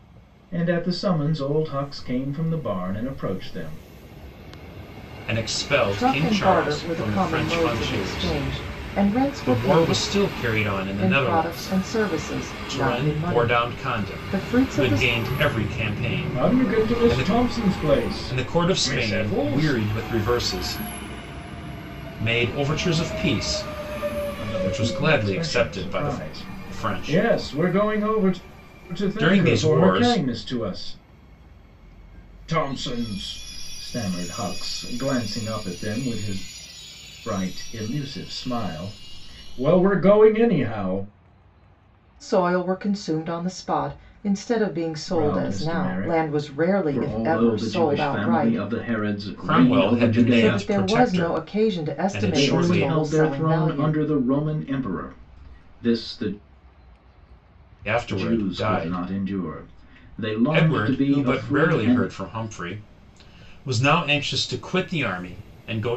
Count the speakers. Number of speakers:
3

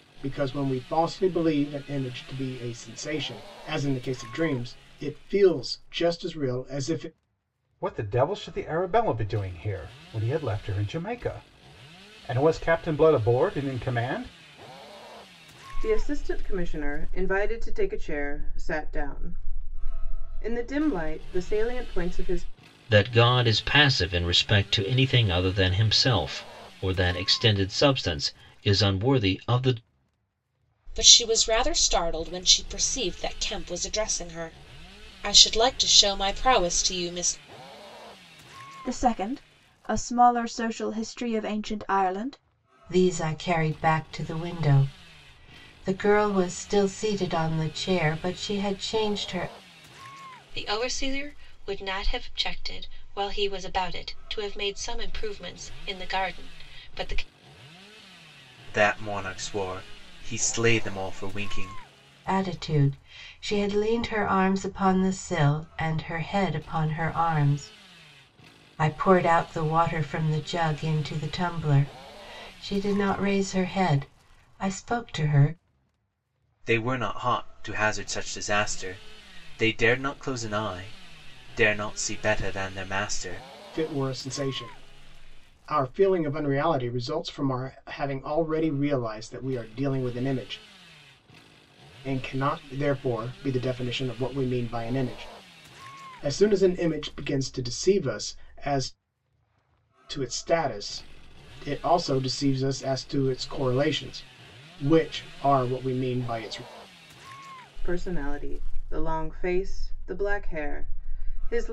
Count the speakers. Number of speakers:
9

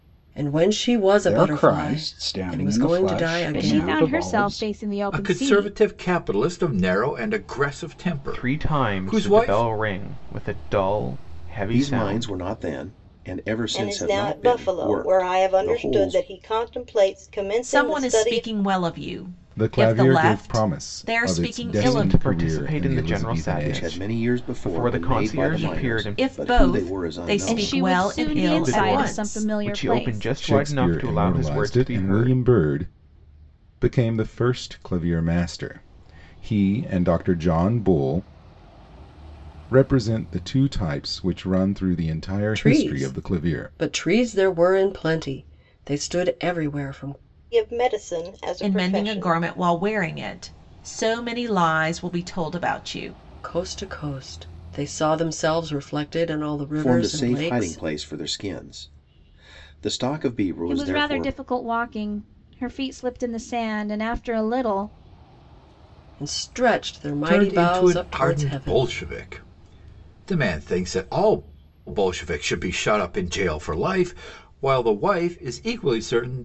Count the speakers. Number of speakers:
9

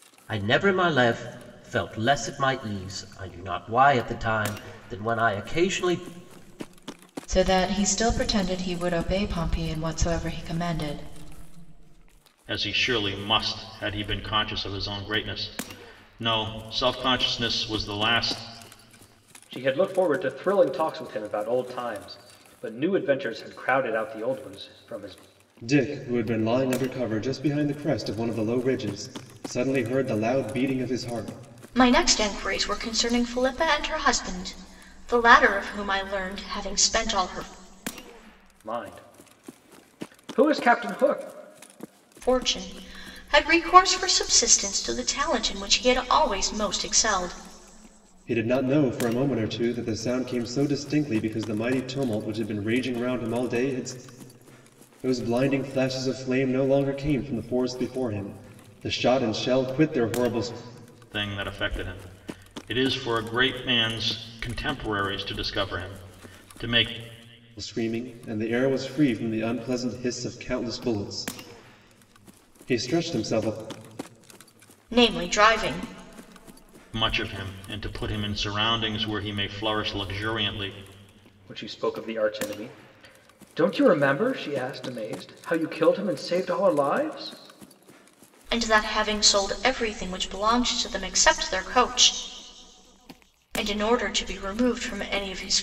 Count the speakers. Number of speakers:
6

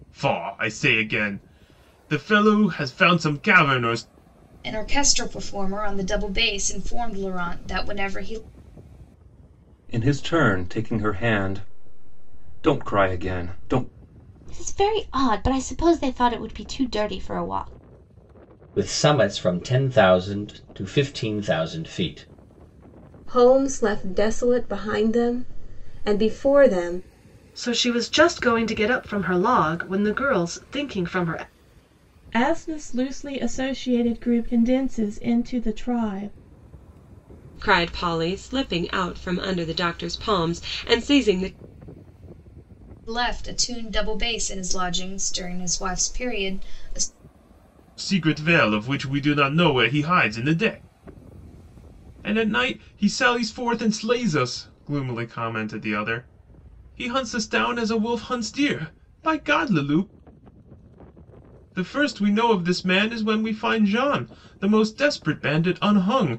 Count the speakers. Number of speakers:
9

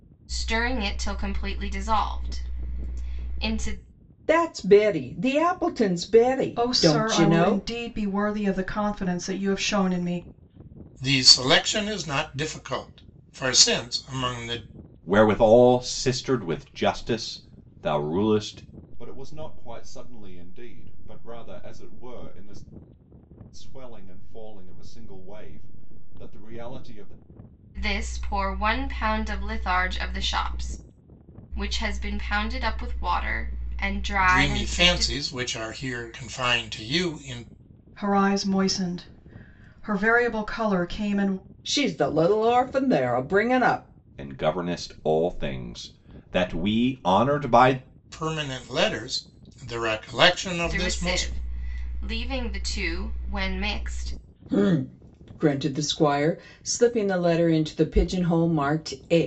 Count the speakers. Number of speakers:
6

